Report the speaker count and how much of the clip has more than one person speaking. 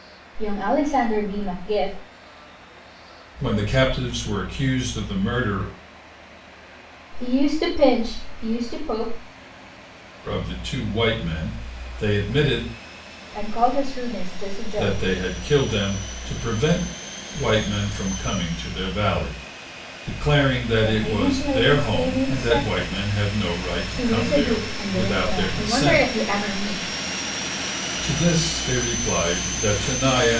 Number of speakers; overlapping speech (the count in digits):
2, about 14%